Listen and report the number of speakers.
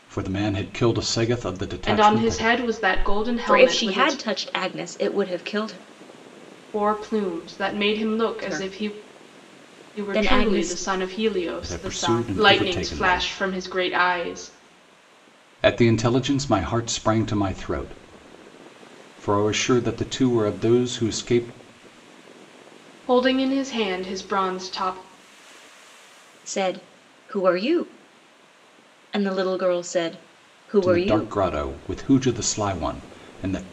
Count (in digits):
3